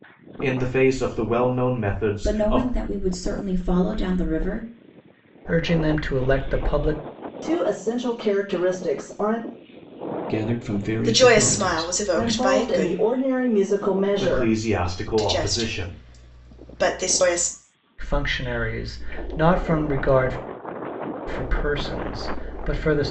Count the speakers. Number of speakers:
6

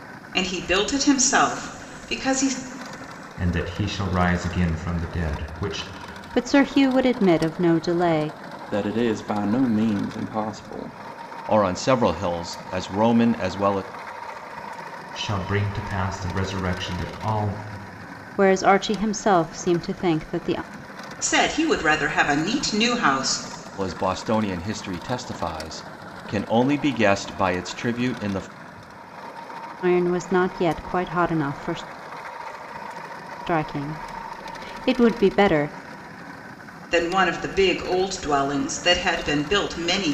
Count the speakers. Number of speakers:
5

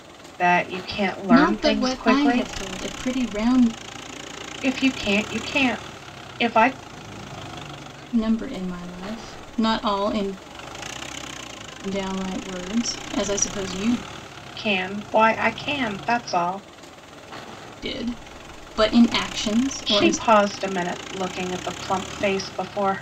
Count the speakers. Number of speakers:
2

